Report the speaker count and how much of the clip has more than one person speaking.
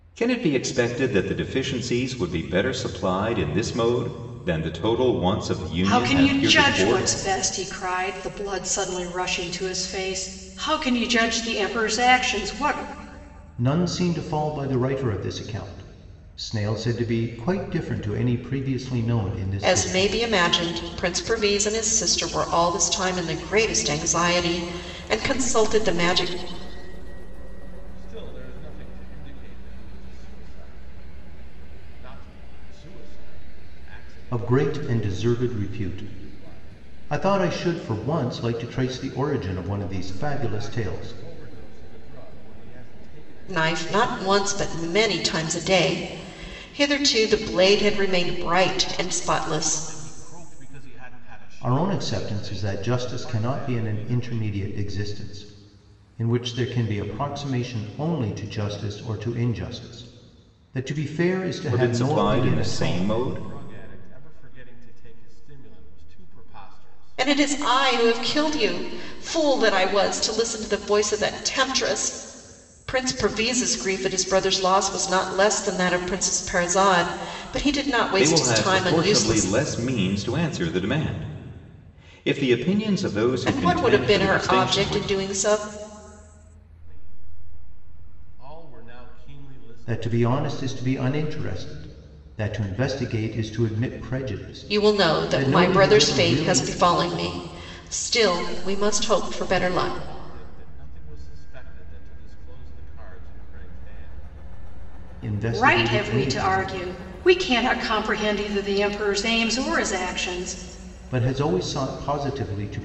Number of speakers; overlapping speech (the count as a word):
five, about 23%